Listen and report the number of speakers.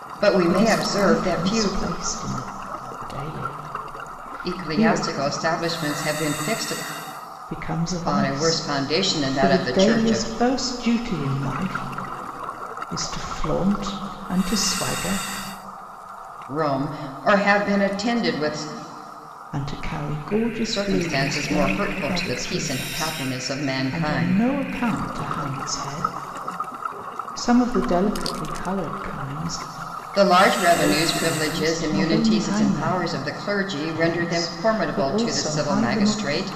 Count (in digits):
2